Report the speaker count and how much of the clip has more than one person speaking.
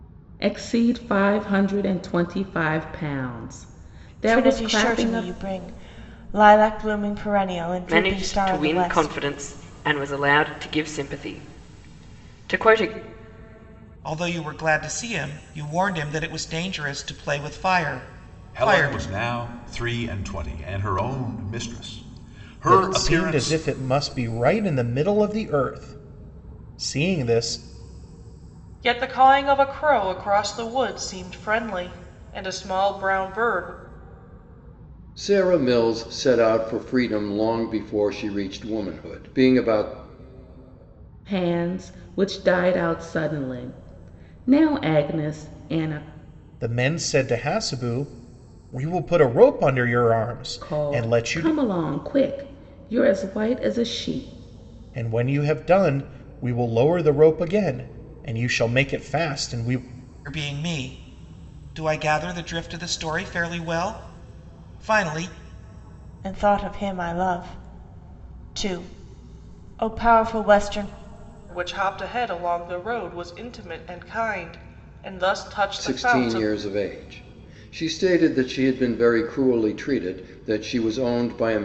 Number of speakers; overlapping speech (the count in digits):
8, about 7%